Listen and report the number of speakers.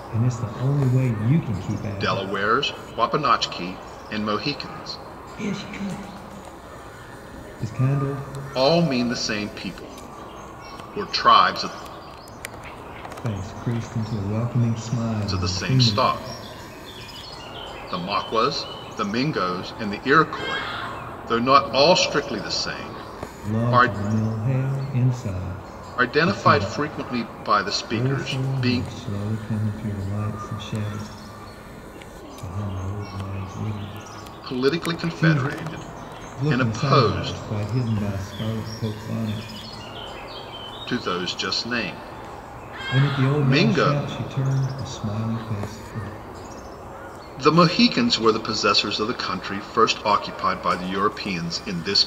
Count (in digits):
2